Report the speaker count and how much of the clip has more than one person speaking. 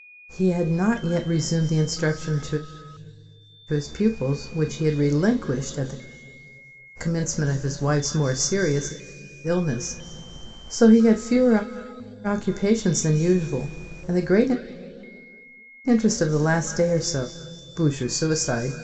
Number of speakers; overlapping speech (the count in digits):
1, no overlap